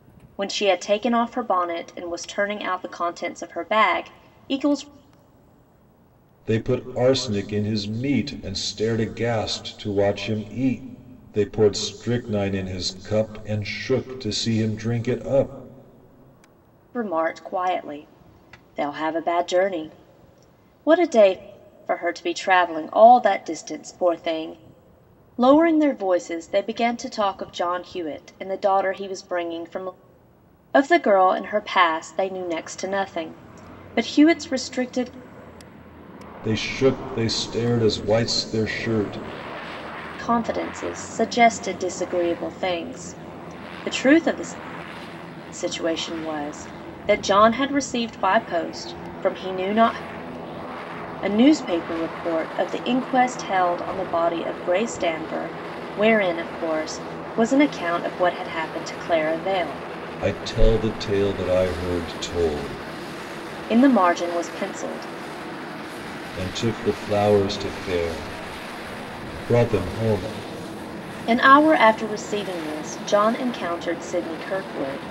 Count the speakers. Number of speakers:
two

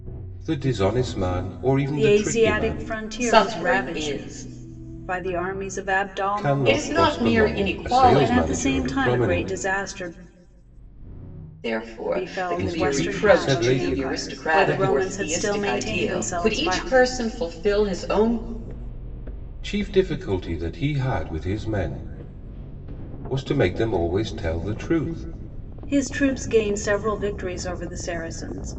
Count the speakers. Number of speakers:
three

